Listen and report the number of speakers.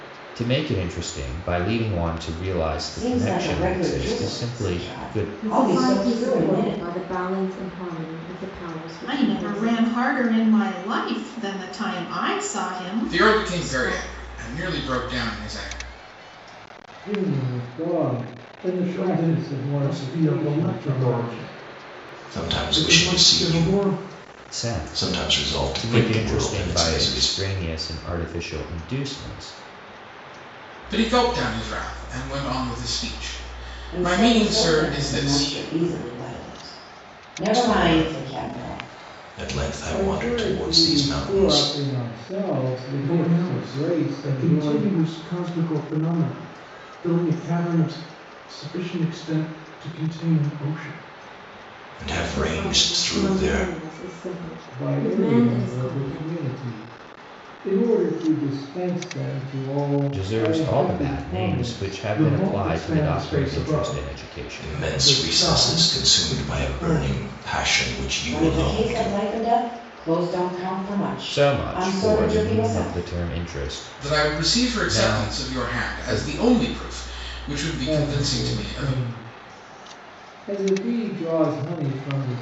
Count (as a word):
eight